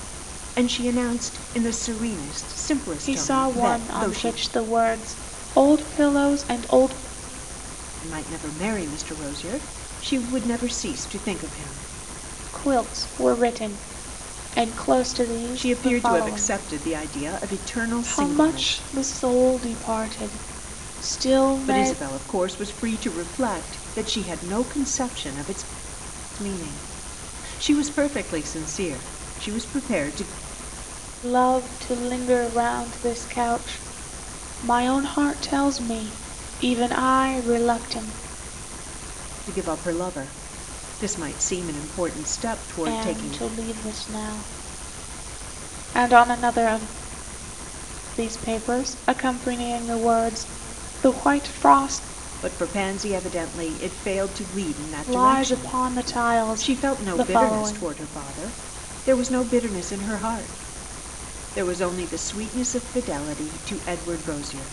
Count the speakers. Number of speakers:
2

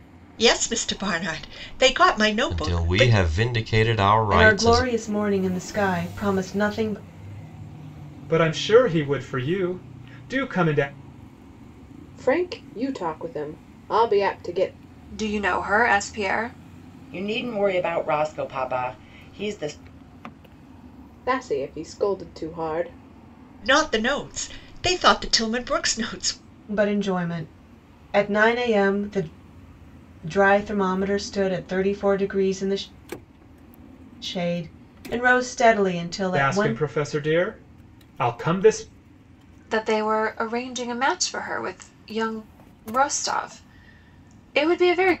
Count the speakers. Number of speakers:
7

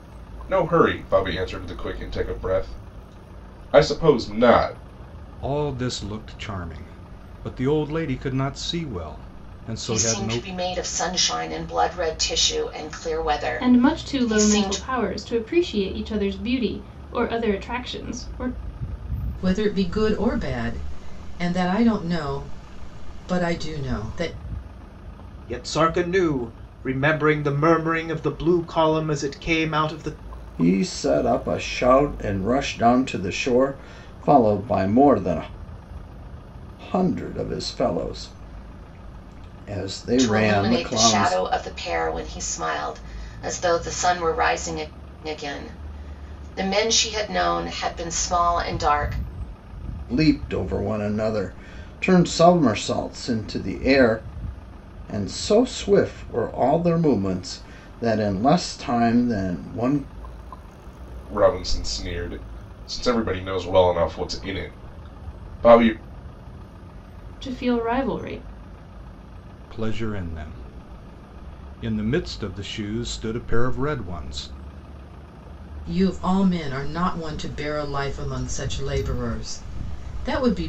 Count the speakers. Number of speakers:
7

